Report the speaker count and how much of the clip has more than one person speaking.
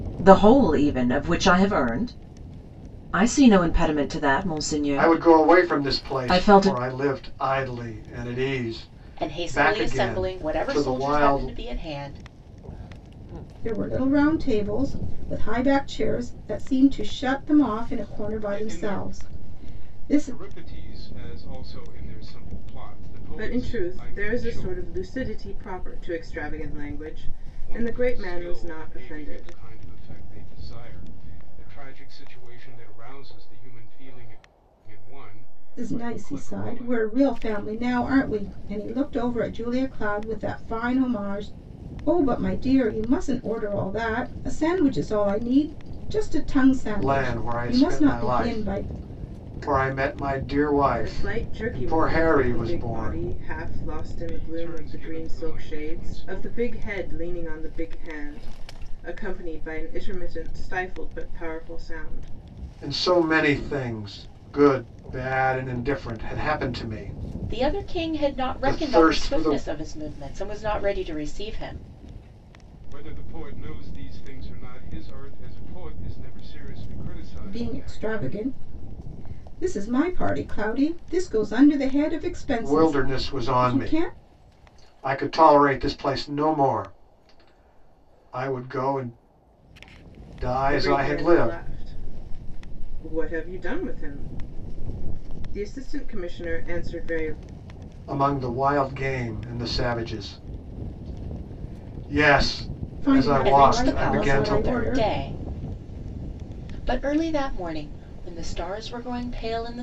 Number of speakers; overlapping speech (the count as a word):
six, about 23%